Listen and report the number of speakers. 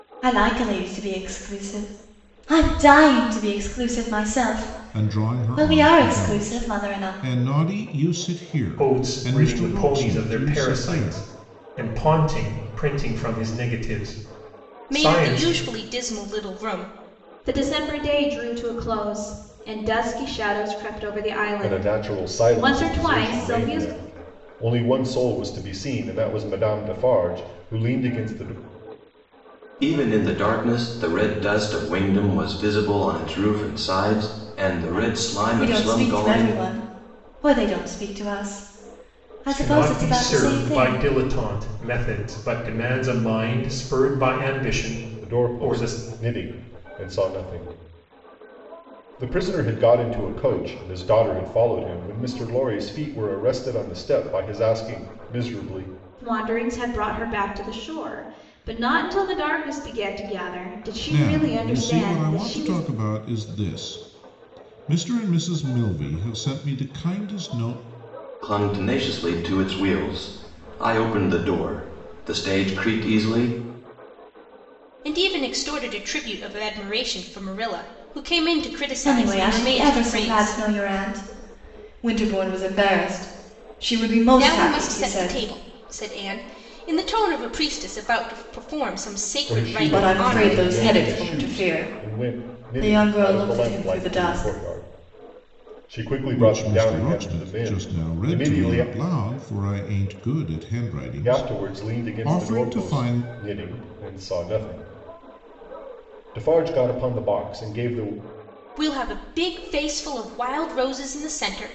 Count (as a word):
seven